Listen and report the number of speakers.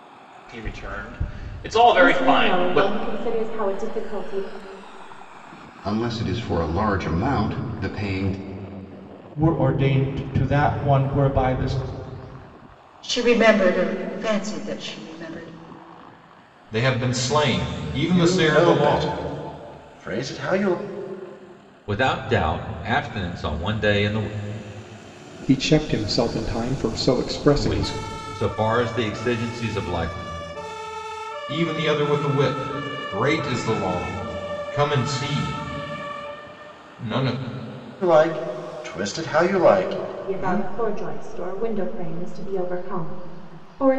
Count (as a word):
nine